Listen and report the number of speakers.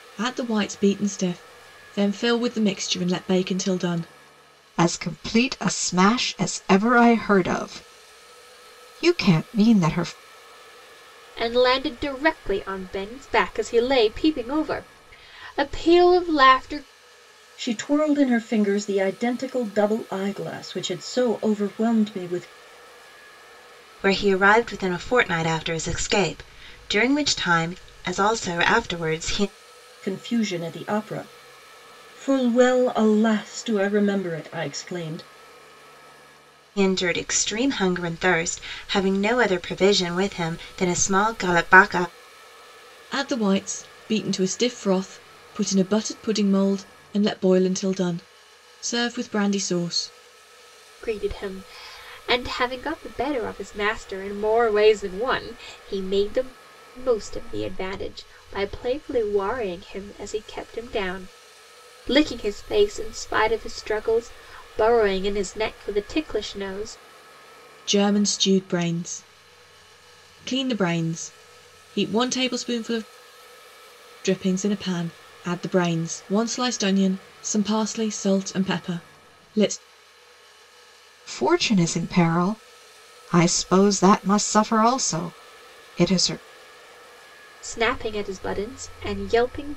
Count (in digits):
5